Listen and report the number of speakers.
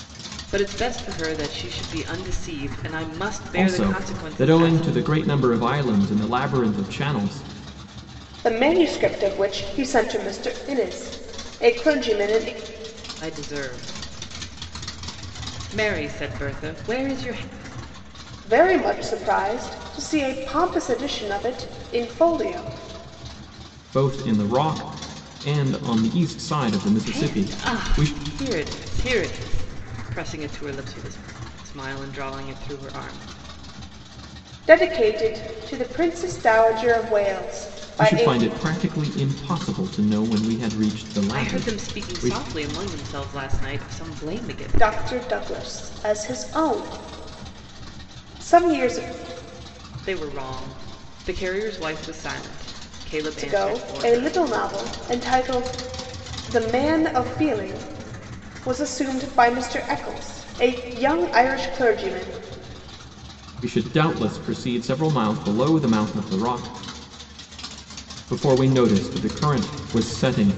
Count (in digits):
3